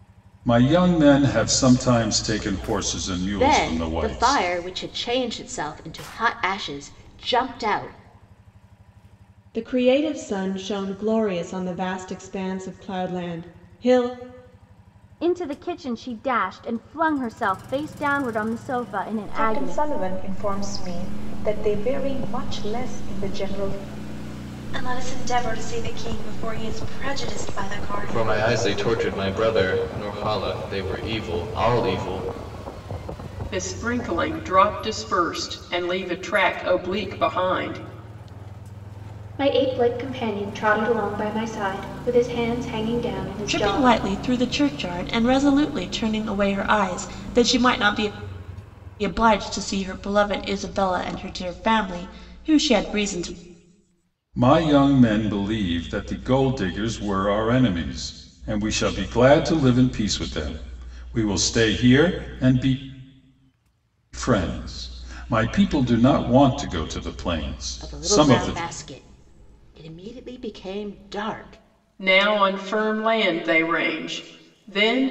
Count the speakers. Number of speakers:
10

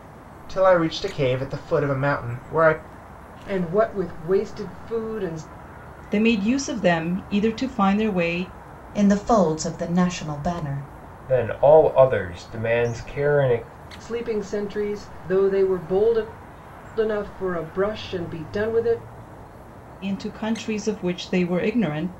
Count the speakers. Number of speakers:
5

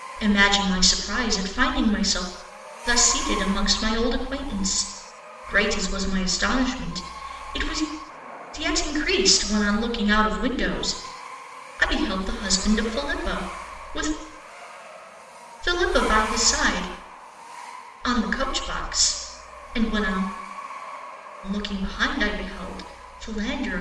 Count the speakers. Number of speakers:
1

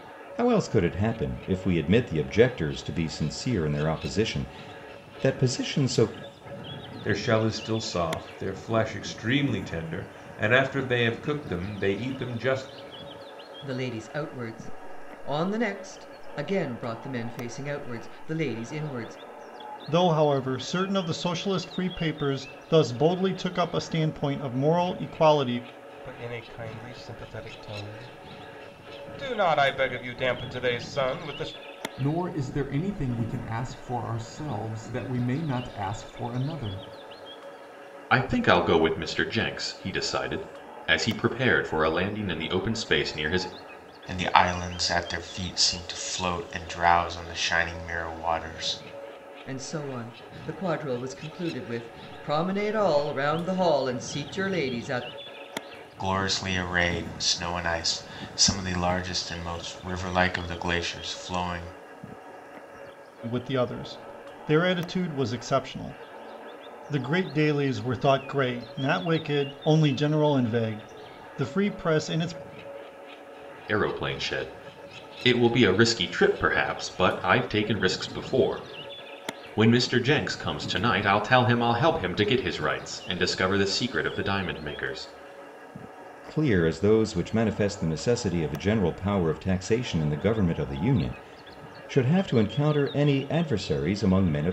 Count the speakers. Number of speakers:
8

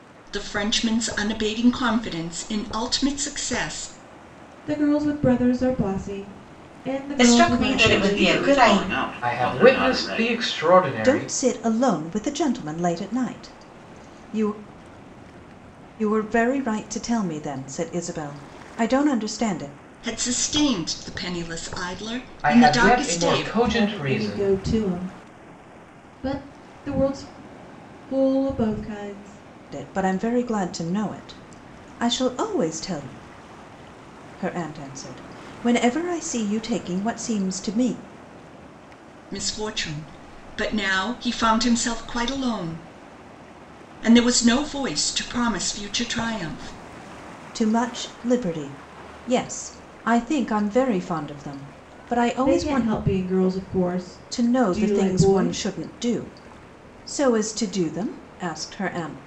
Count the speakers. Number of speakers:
6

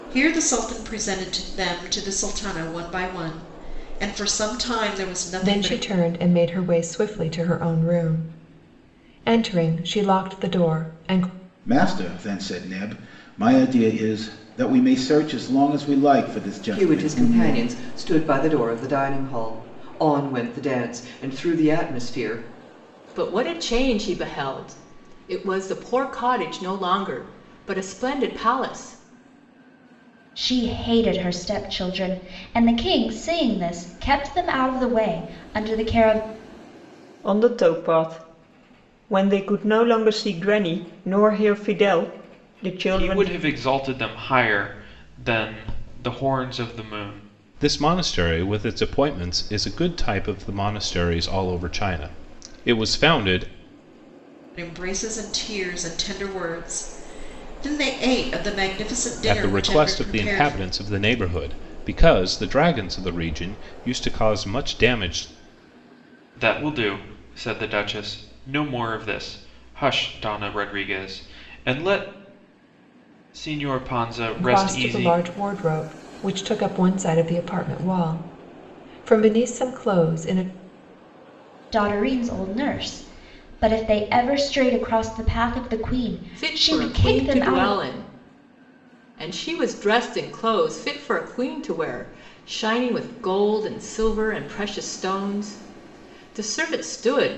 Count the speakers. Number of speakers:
9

